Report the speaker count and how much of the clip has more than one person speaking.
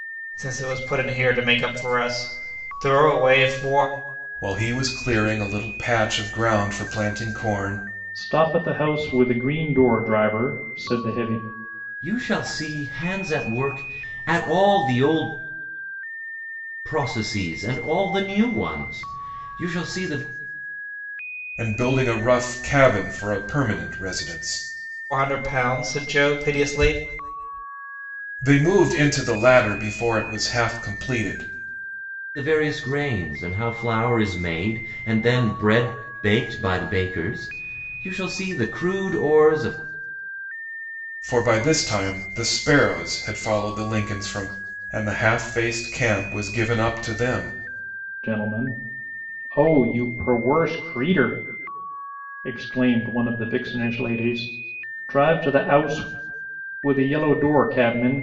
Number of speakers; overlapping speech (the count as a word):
four, no overlap